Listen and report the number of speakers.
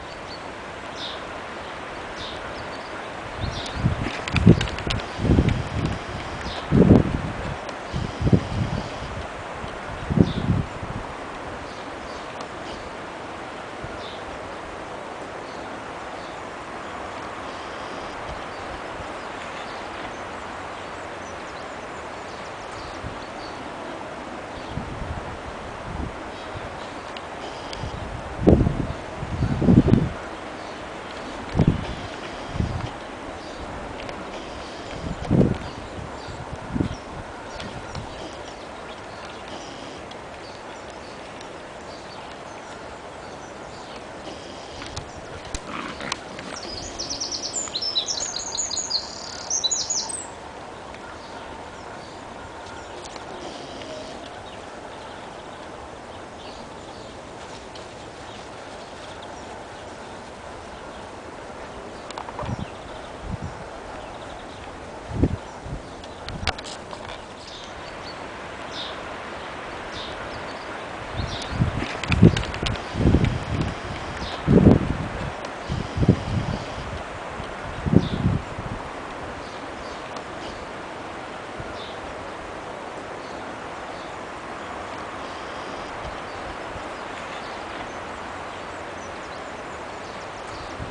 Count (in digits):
0